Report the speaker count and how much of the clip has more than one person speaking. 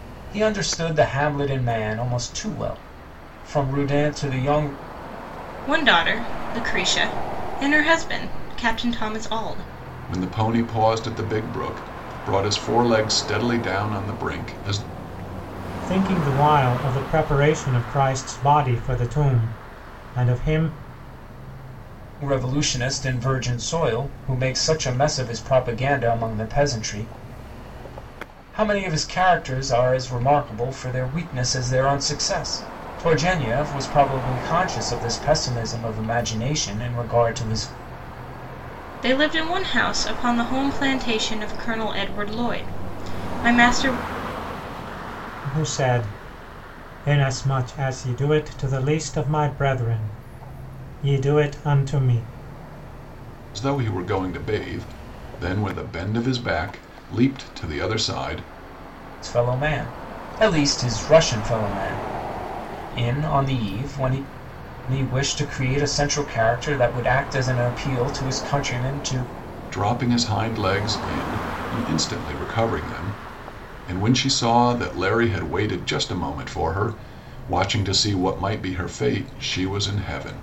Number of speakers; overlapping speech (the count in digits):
4, no overlap